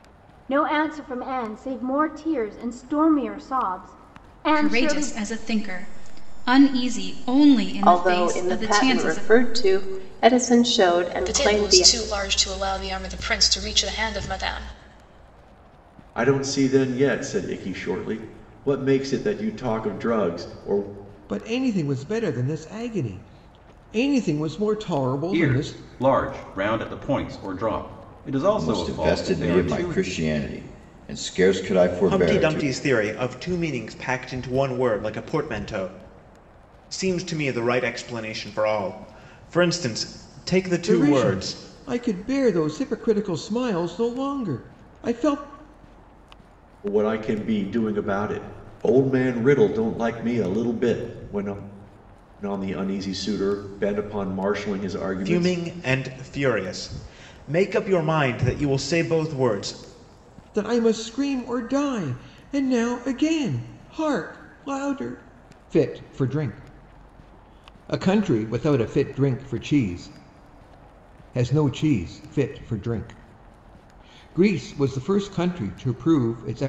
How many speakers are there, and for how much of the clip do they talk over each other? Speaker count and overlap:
nine, about 9%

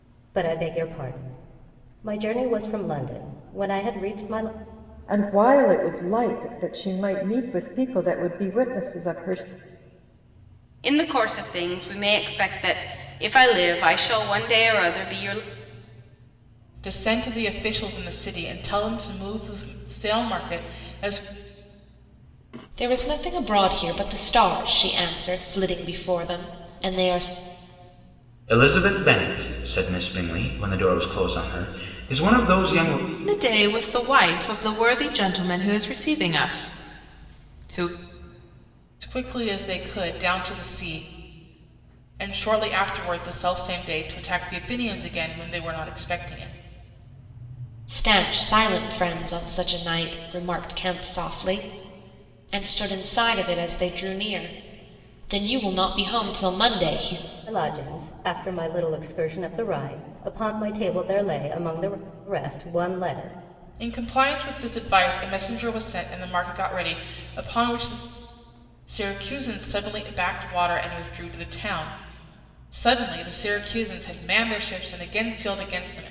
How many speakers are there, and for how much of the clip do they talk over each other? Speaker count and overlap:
seven, no overlap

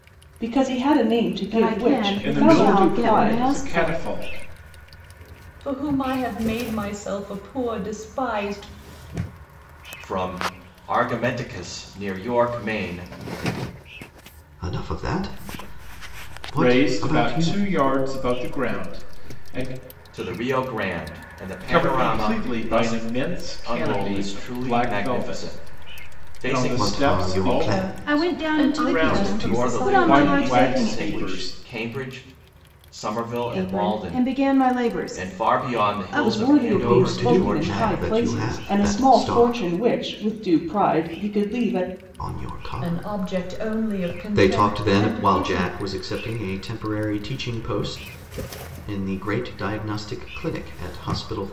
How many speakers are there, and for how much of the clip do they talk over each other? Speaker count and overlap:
six, about 41%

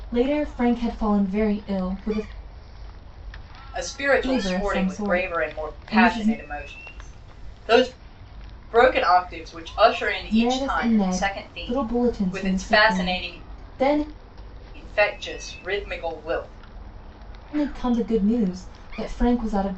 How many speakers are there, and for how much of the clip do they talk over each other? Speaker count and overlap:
two, about 26%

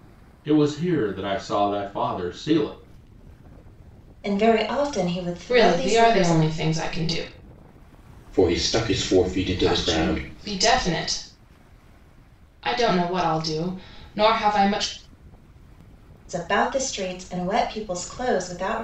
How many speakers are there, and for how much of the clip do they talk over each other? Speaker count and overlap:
four, about 9%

